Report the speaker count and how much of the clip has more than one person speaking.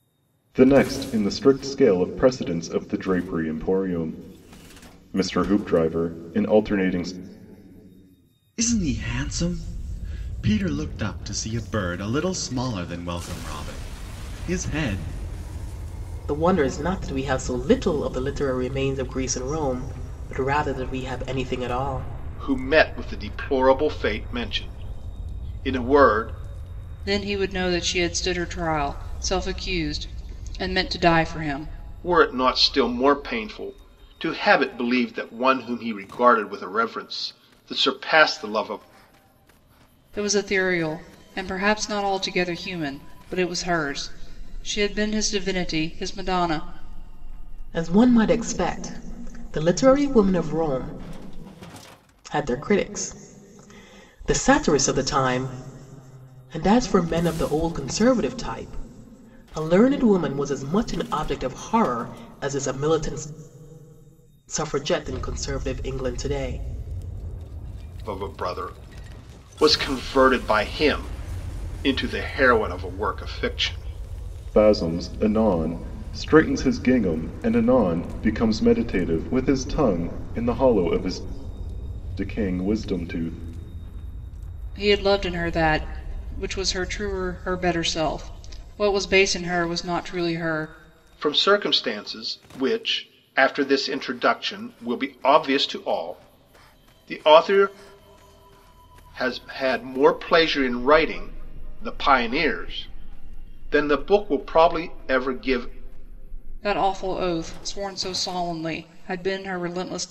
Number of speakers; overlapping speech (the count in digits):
5, no overlap